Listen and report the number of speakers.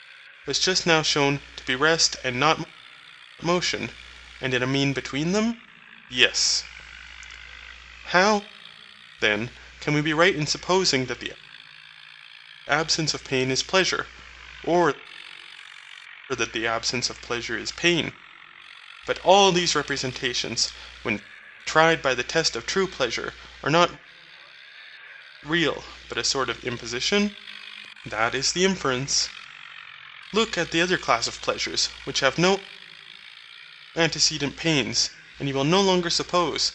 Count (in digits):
1